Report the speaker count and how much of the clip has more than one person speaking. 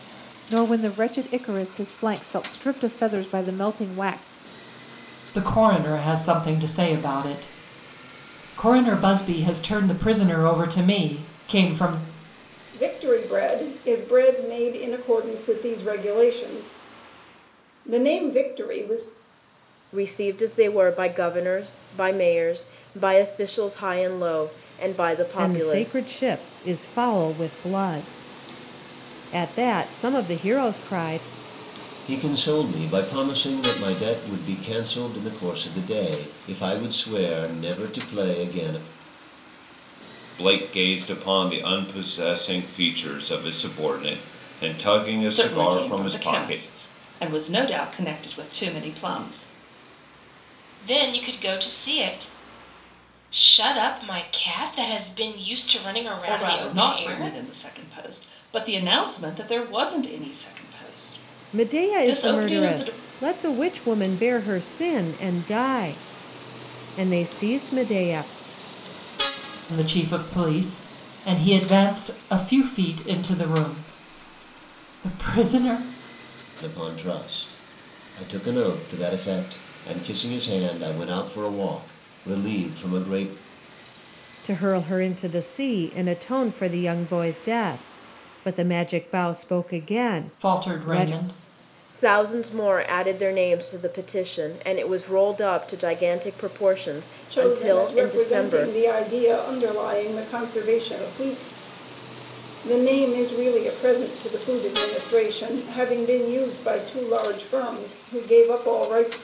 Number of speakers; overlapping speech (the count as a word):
nine, about 6%